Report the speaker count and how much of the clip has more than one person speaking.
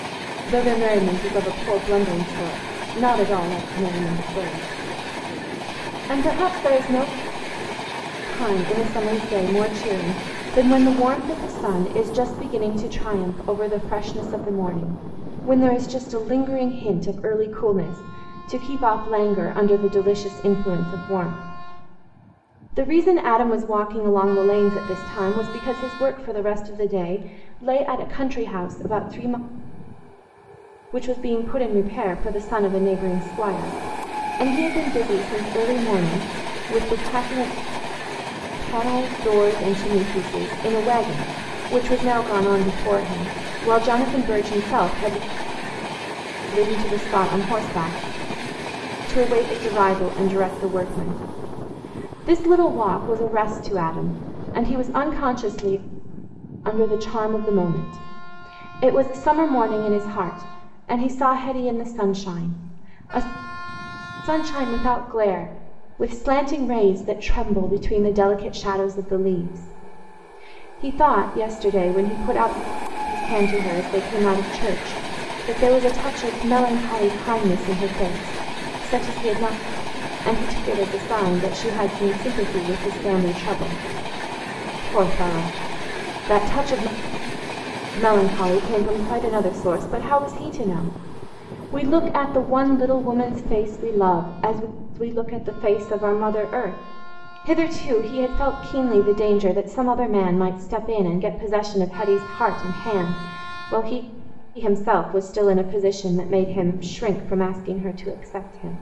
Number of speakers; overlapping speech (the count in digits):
1, no overlap